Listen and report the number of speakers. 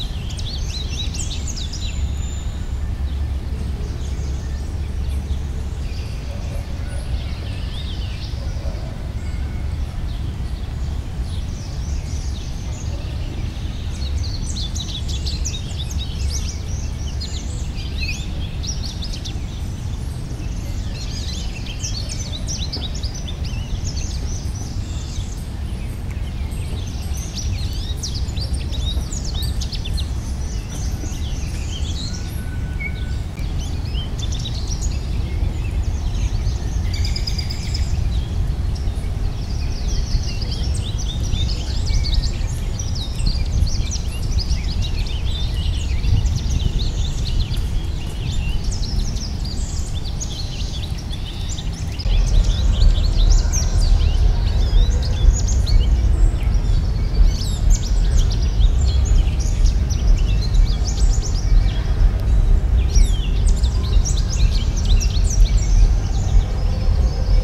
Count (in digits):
0